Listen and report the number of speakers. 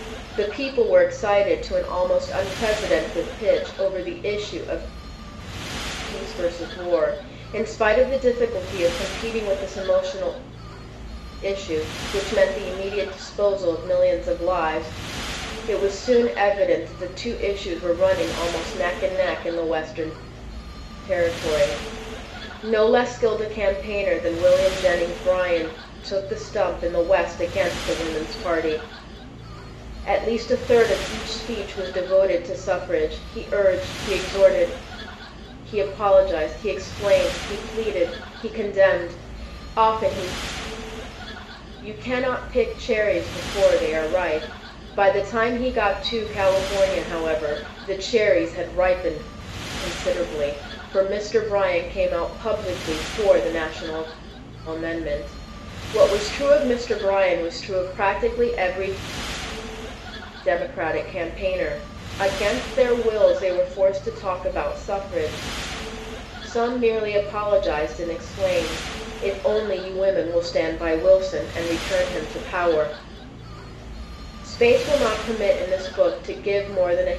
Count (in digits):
1